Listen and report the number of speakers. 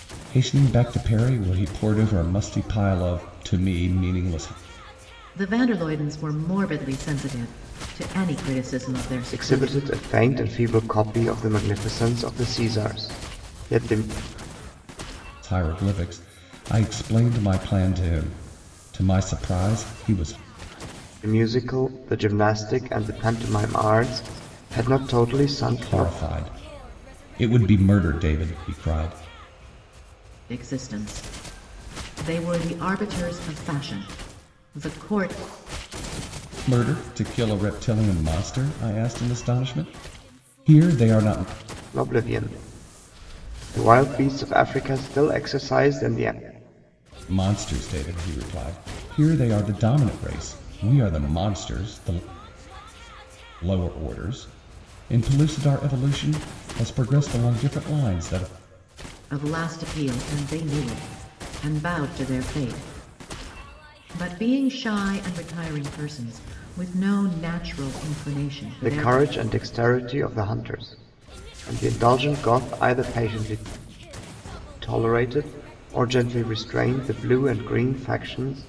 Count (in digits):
3